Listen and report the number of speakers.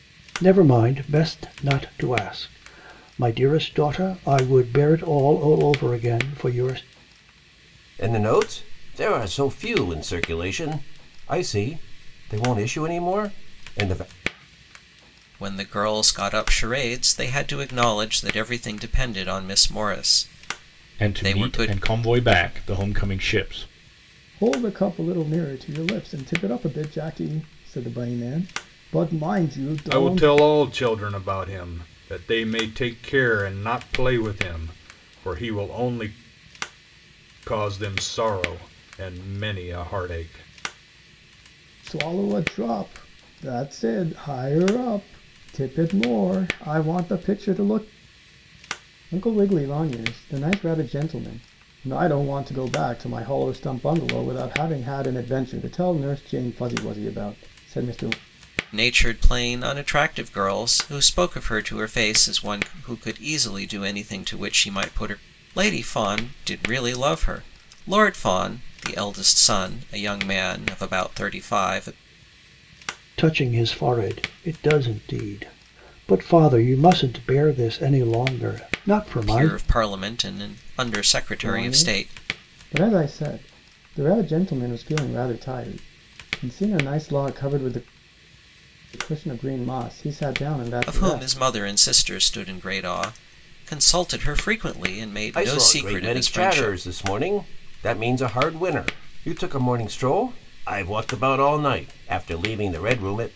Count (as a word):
six